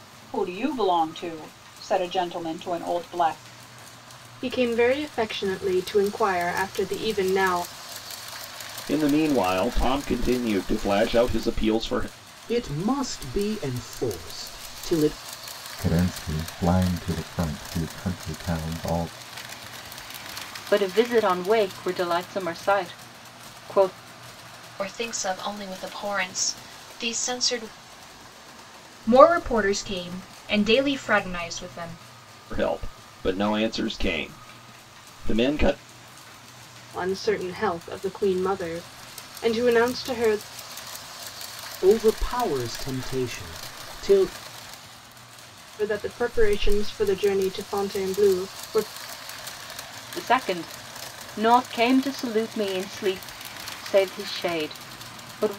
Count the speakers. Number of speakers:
8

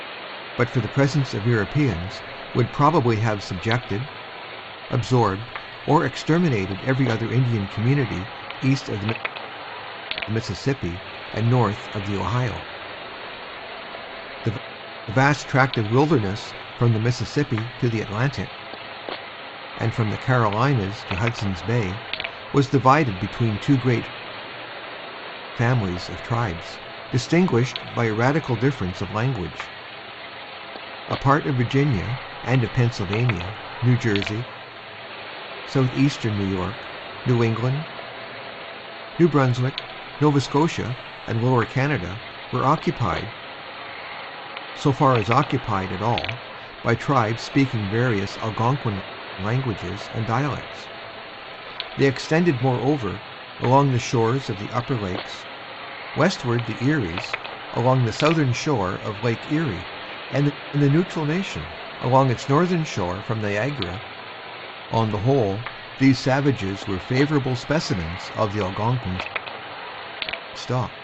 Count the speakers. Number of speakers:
1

